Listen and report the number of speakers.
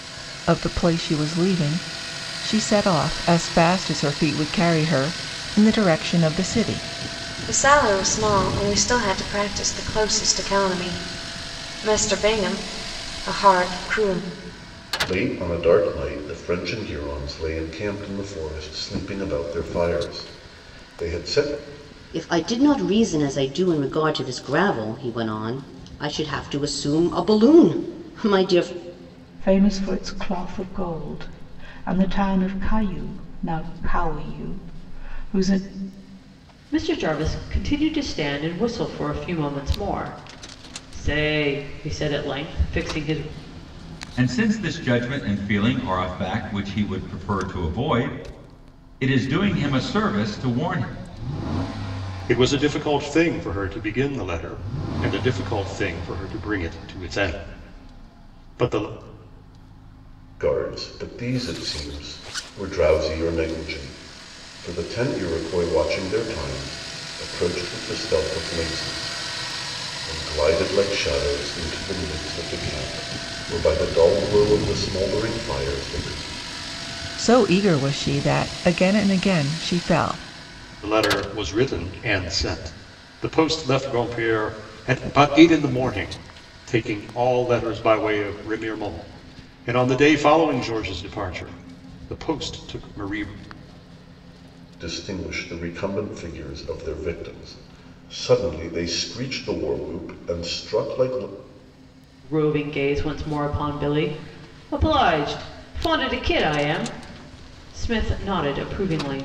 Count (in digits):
8